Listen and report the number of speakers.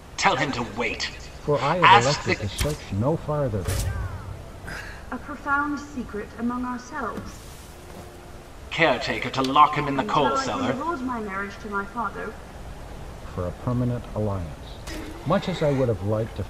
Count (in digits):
3